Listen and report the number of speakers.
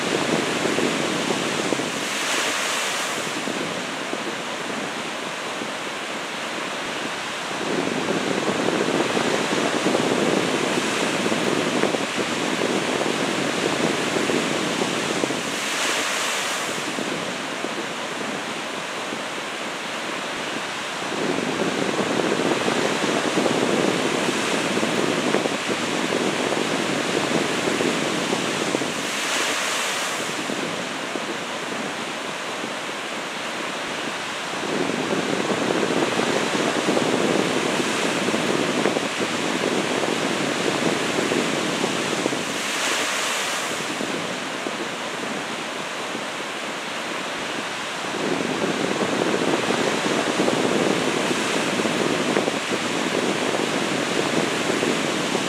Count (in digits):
0